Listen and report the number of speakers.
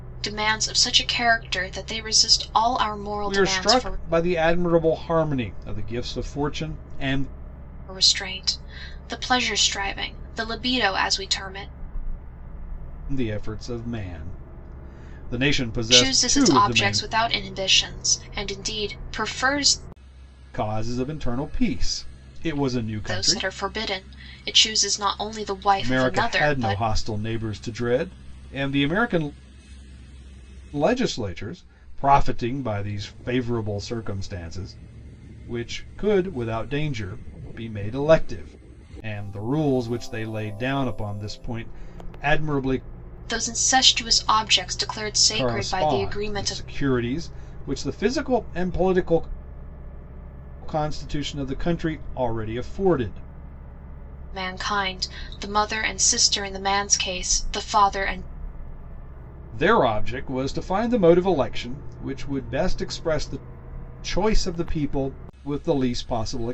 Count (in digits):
2